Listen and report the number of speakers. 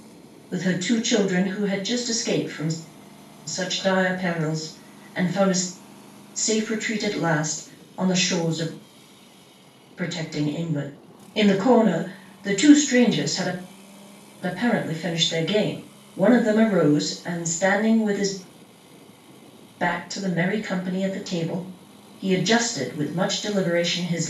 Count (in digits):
1